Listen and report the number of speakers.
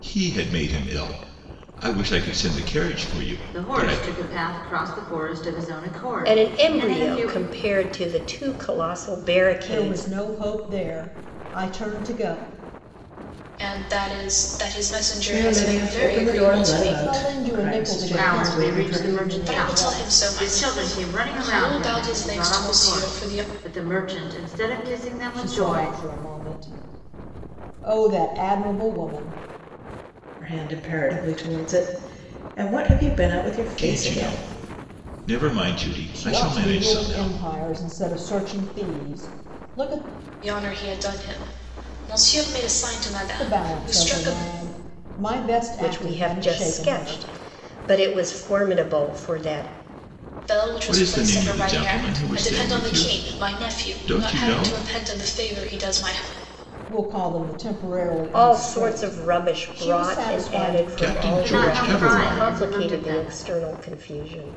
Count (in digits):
6